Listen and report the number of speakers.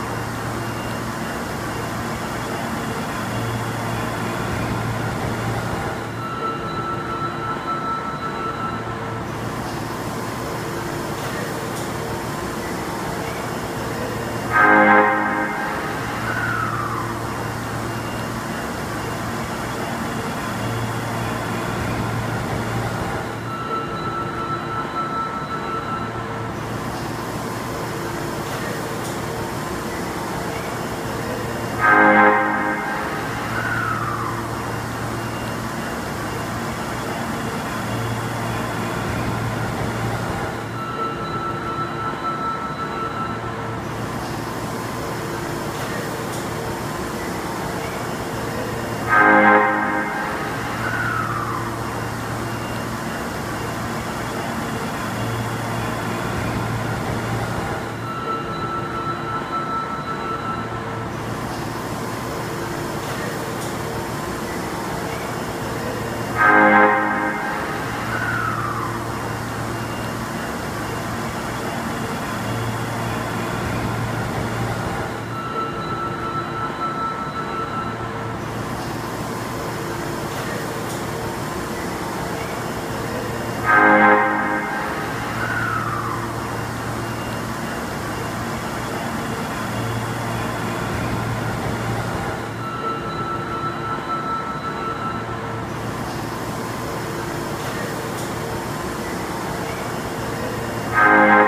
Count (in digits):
0